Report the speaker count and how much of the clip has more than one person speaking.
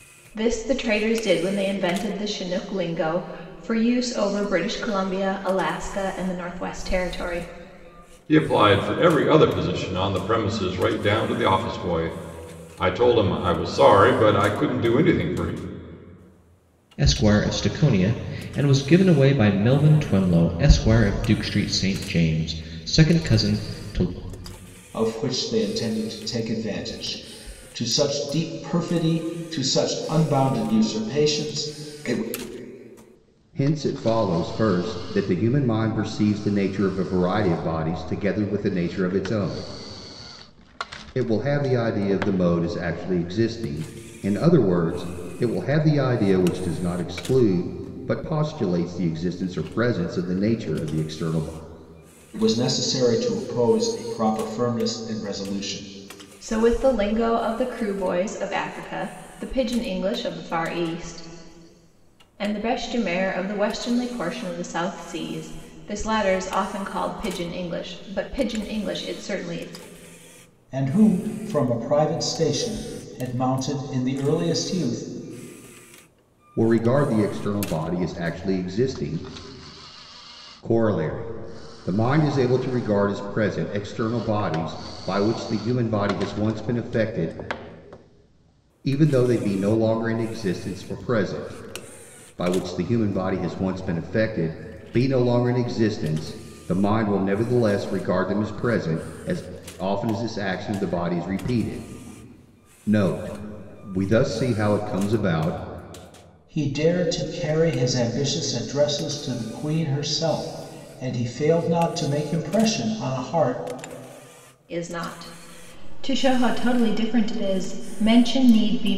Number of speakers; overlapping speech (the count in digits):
5, no overlap